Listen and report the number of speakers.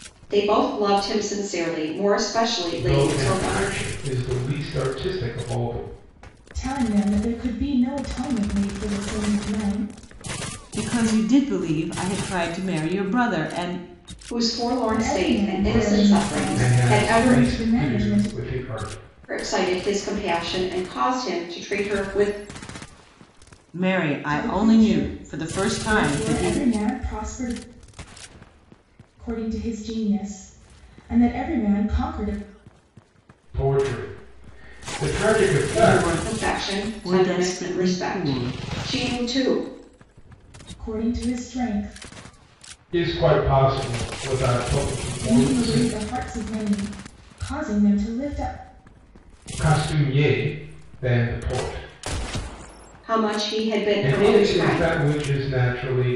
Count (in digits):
4